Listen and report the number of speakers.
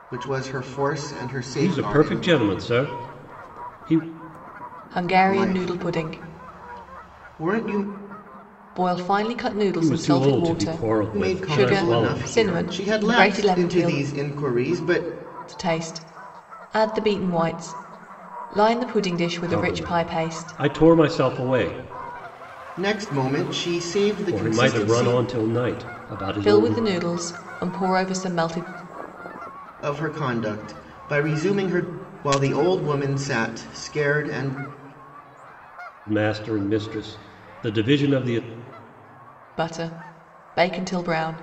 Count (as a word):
three